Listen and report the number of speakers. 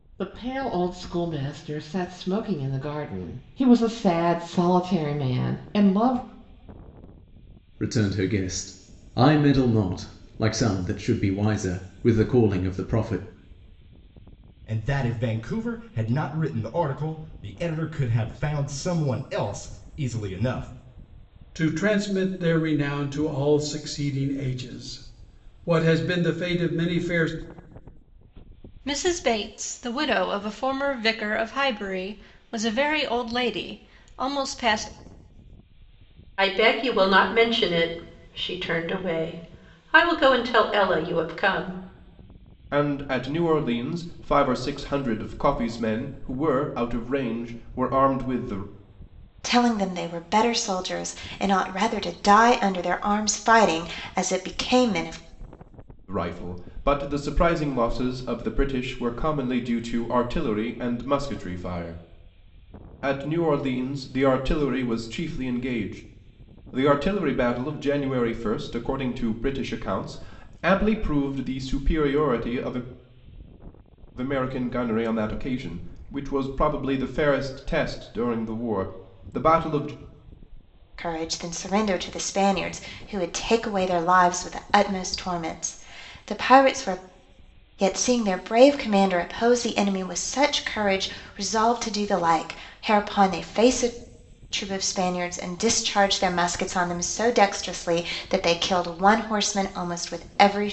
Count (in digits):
8